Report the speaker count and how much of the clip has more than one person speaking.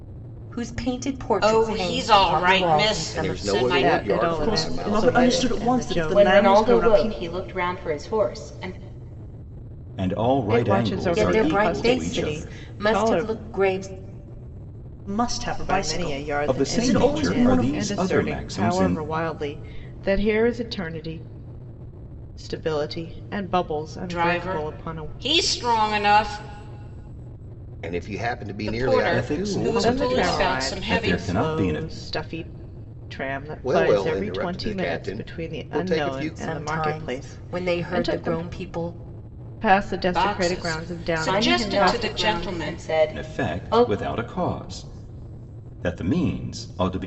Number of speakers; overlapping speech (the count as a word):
seven, about 52%